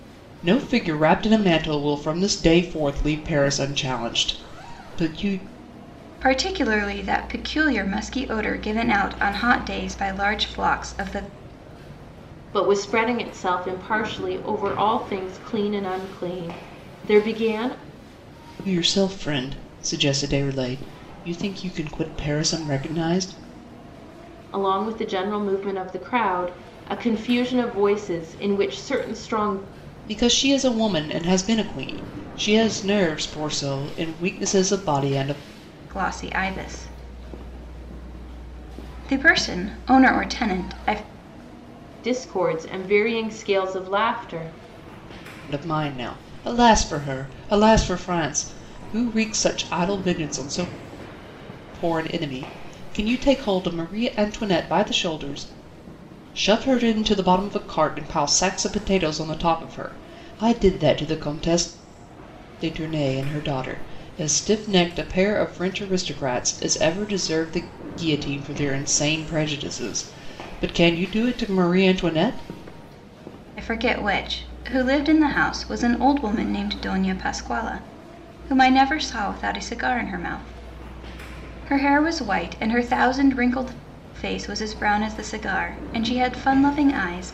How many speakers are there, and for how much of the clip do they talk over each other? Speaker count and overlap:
3, no overlap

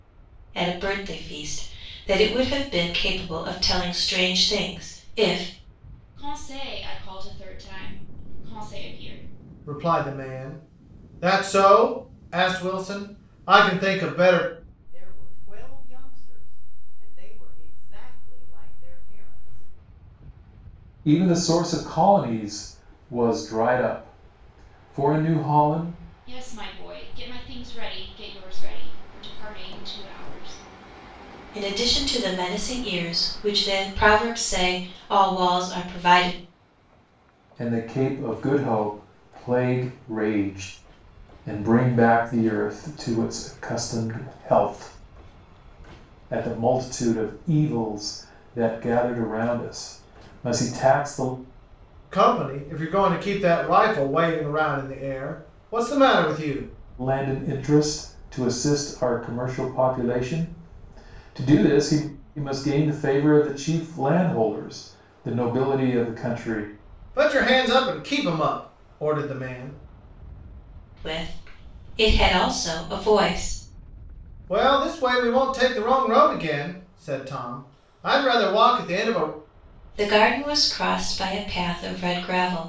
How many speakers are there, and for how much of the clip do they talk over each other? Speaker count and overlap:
5, no overlap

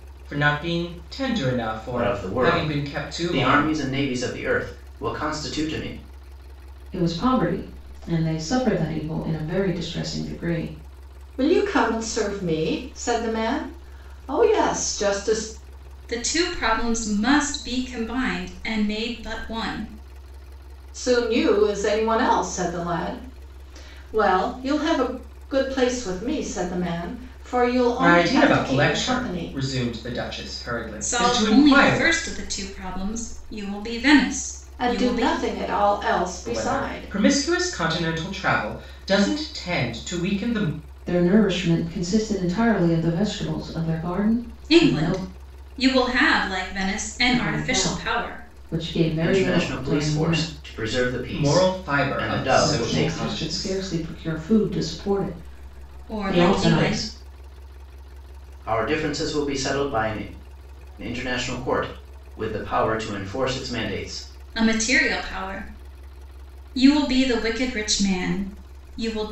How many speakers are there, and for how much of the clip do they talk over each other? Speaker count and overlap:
5, about 18%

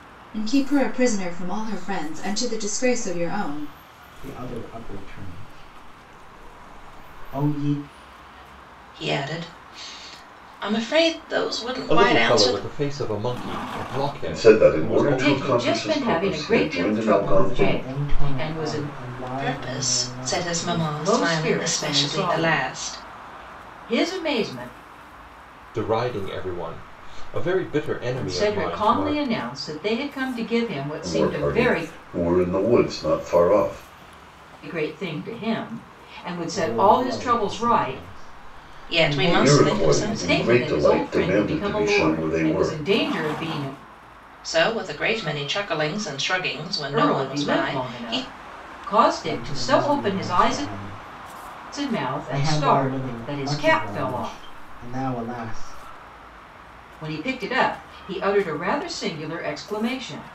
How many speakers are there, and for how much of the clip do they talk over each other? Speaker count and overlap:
6, about 36%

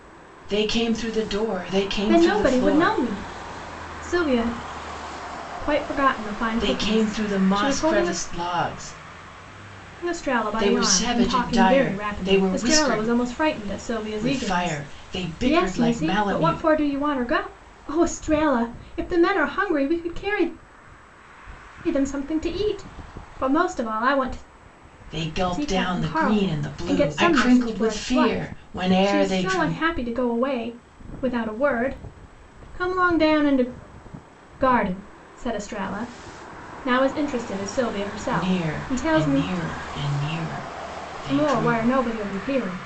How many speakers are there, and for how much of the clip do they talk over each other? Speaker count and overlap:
2, about 31%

